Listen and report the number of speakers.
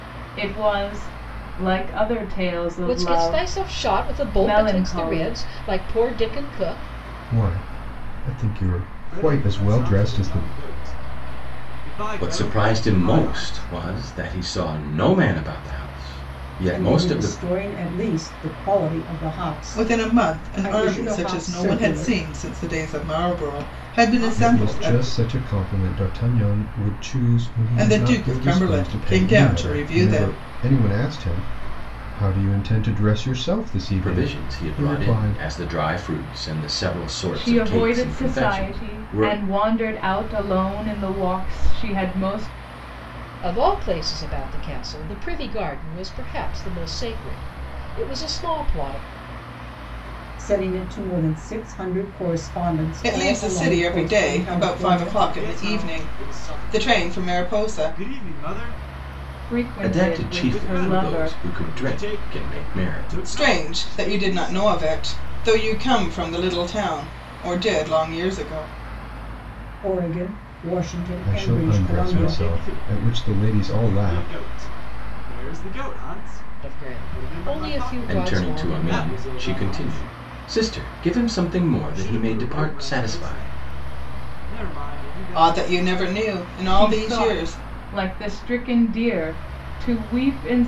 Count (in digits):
7